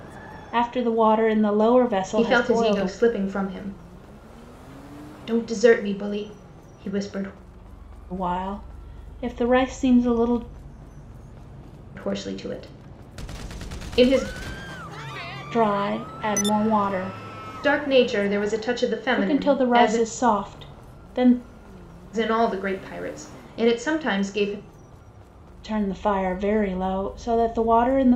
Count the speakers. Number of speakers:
2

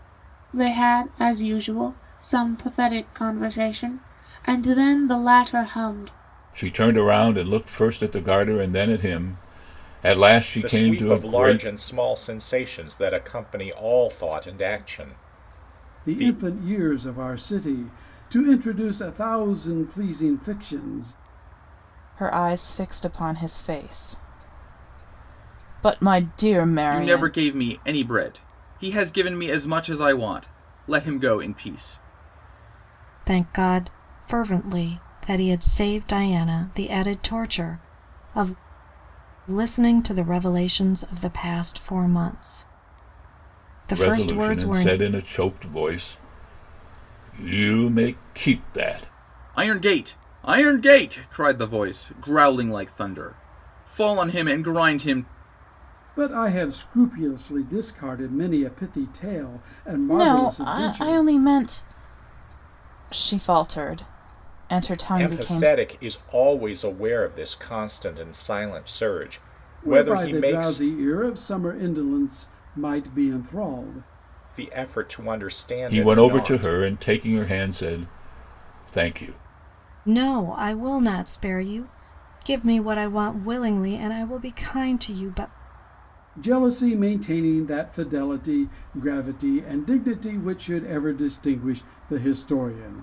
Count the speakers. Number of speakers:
7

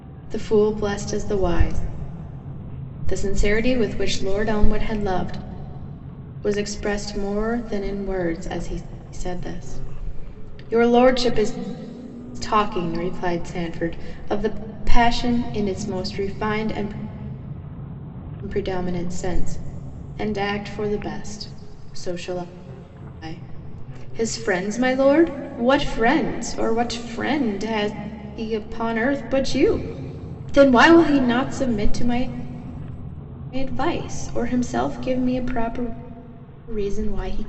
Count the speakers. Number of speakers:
1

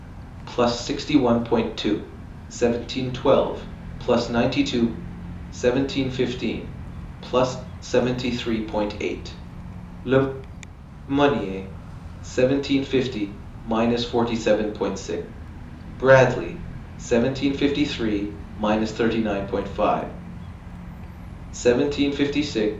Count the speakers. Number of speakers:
1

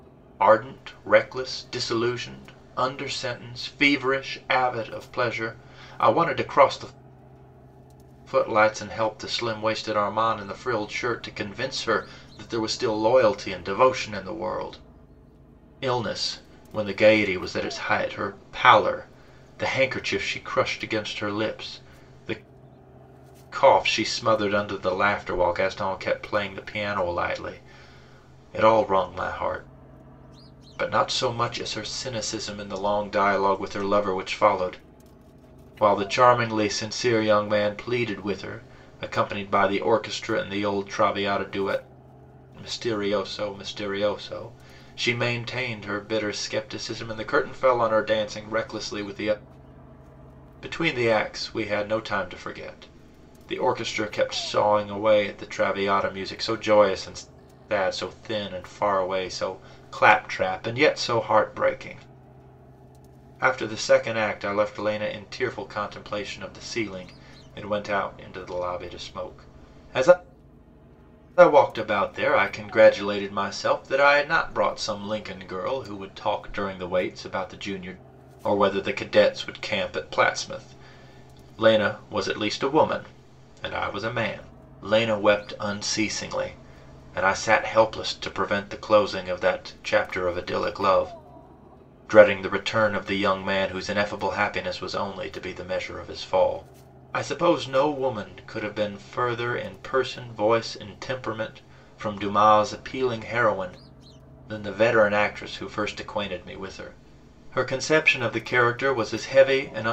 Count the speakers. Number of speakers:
1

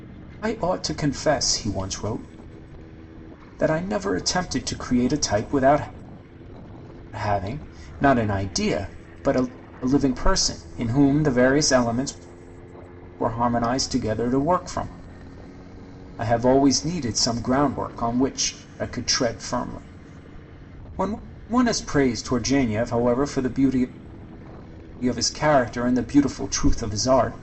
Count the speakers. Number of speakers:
1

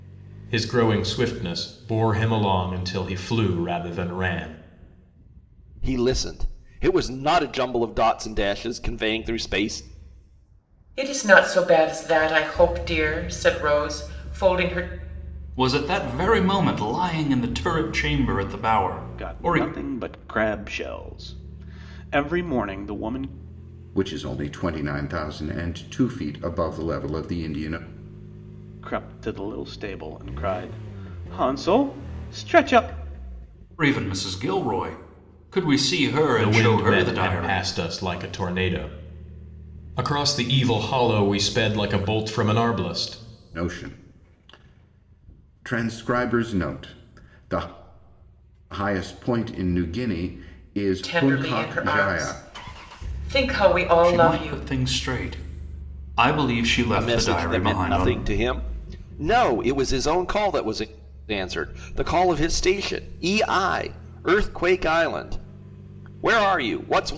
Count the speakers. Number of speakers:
6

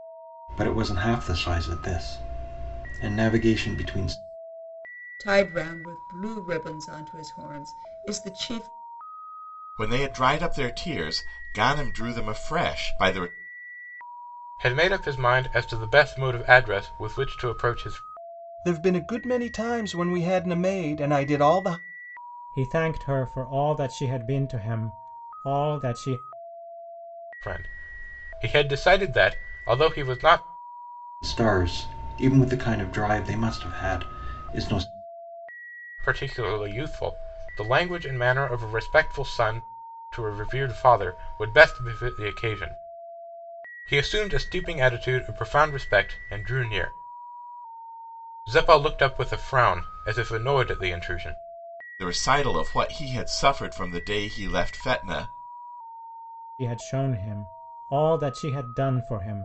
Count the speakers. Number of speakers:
6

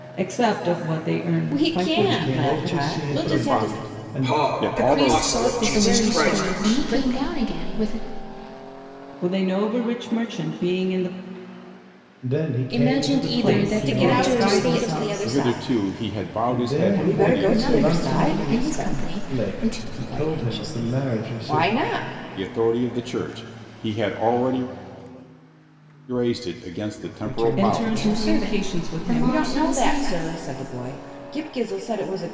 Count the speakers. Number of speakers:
7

